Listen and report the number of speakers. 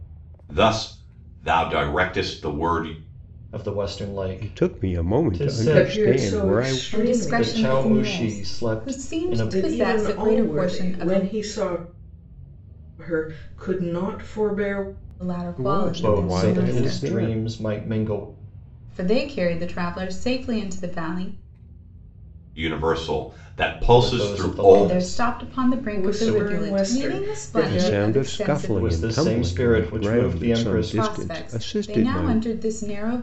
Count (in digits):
5